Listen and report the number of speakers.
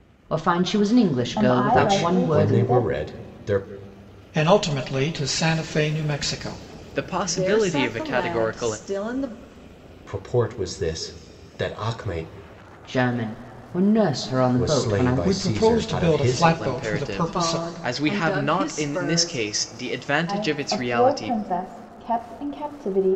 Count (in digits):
6